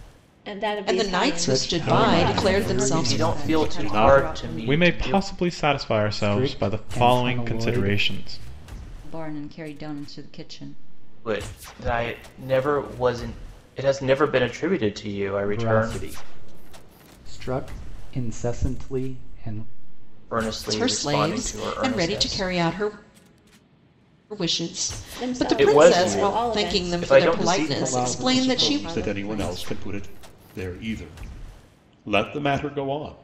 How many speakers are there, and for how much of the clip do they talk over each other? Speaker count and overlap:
seven, about 39%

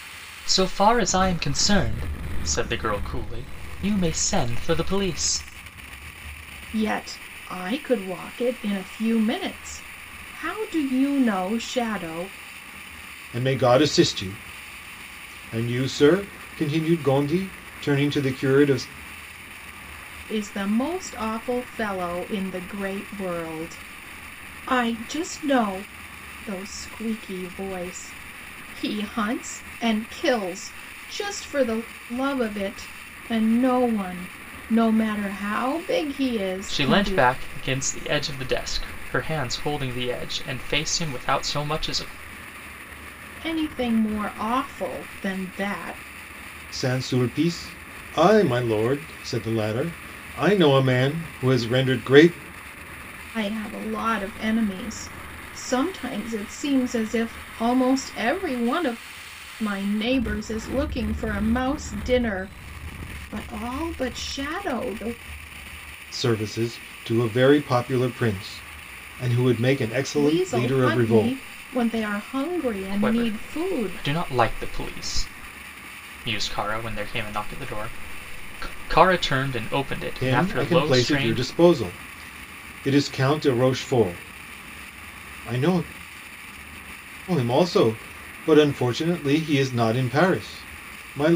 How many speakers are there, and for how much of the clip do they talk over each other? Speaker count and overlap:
three, about 5%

